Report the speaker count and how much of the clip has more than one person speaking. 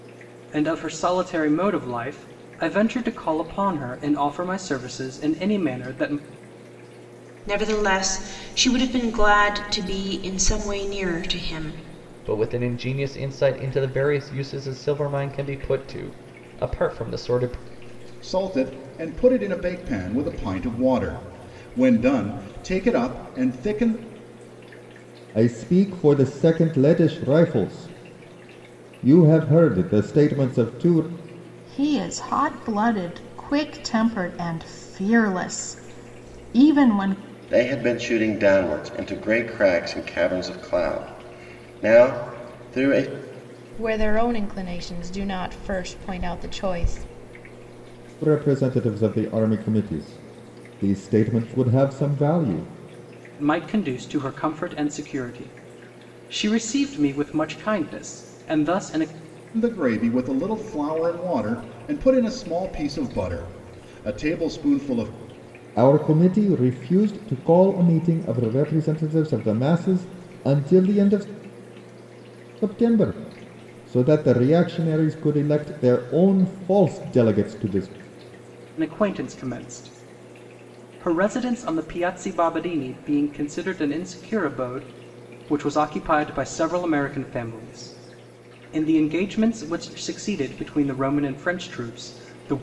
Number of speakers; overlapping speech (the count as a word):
eight, no overlap